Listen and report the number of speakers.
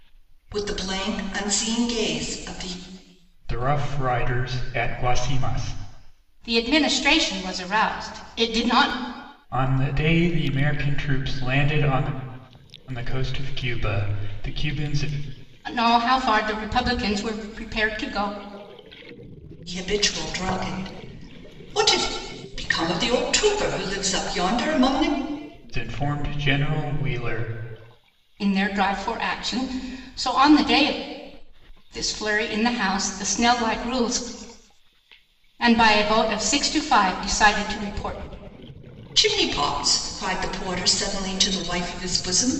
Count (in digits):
3